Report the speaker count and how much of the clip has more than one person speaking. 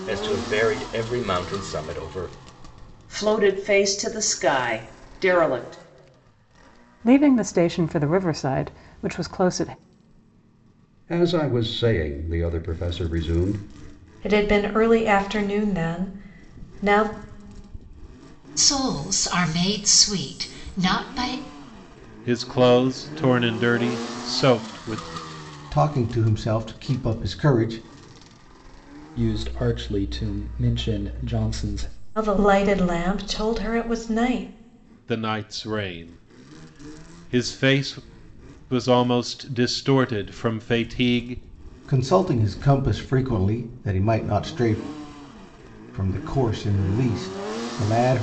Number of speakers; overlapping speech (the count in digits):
9, no overlap